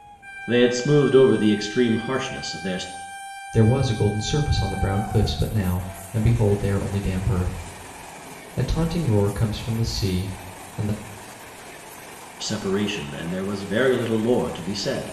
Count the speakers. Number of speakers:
two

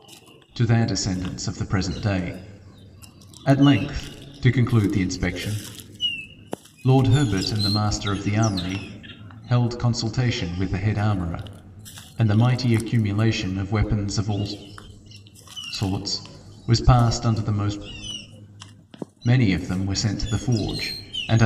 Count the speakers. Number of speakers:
one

